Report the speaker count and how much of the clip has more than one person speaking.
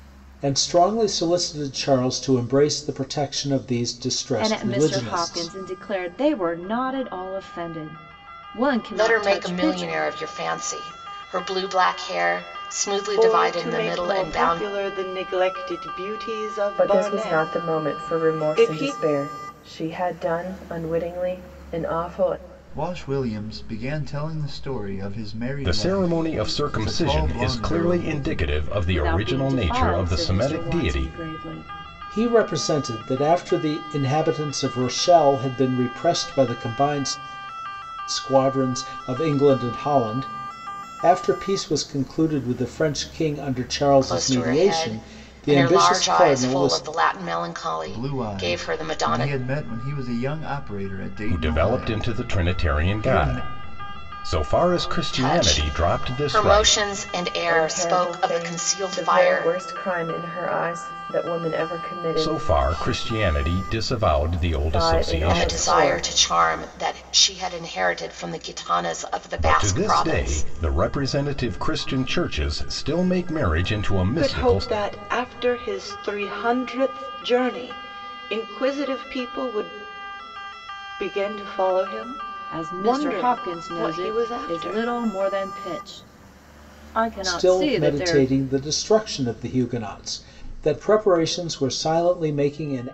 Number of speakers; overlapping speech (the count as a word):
seven, about 31%